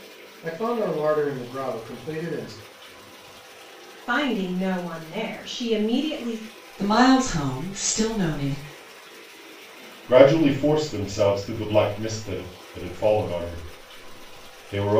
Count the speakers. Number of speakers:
4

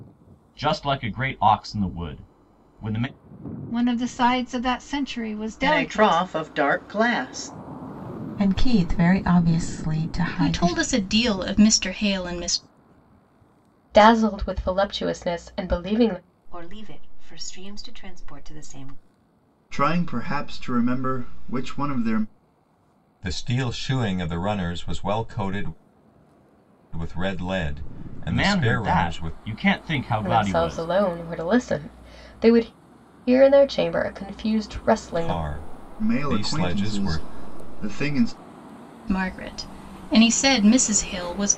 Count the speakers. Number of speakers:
9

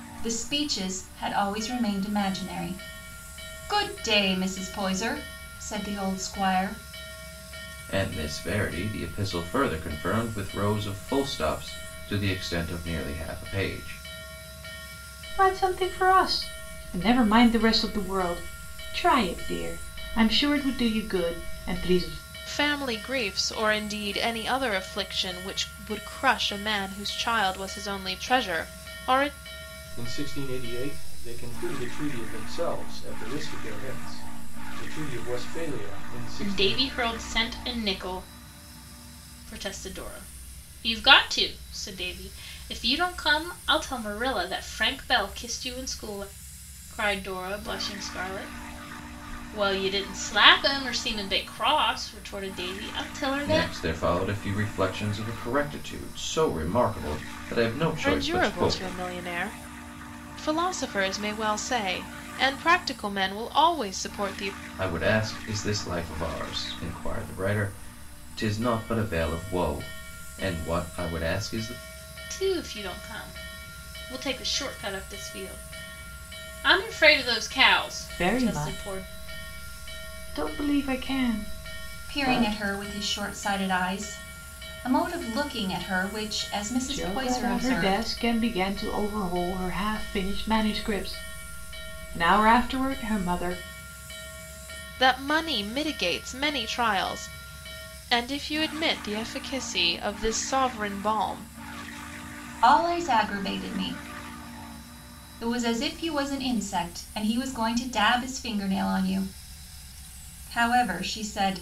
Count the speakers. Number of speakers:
6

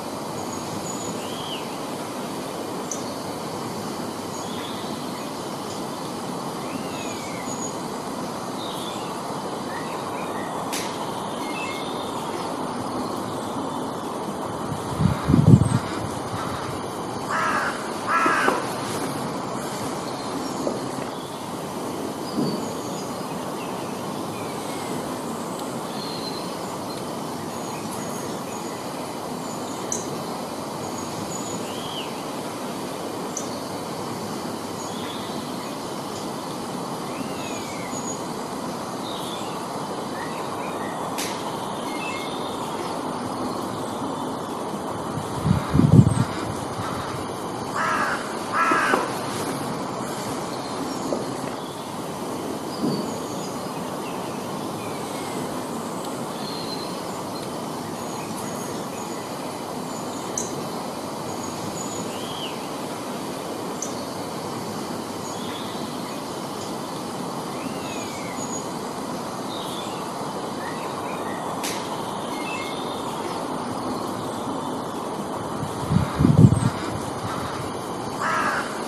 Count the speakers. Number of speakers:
0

